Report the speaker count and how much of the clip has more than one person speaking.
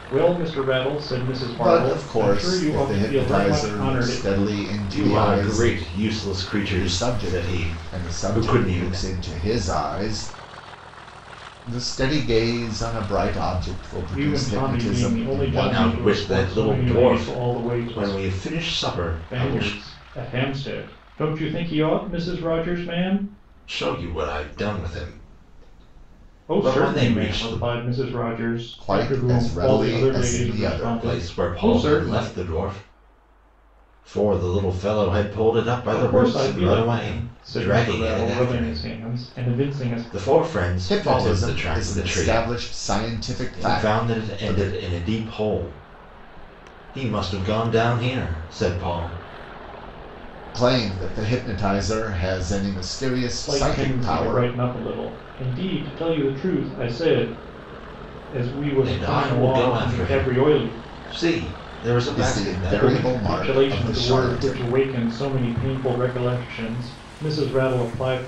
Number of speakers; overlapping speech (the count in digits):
3, about 41%